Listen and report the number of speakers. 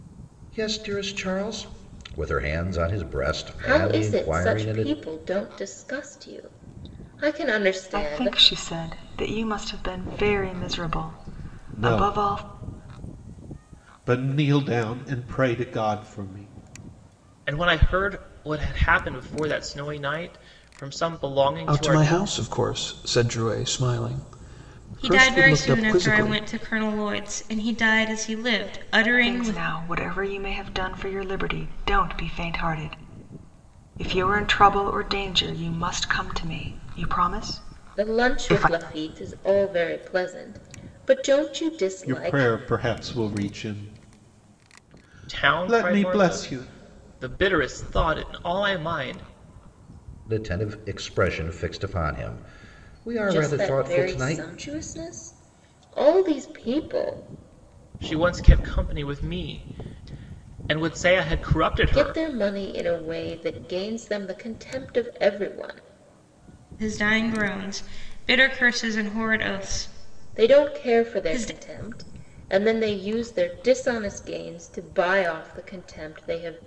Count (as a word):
seven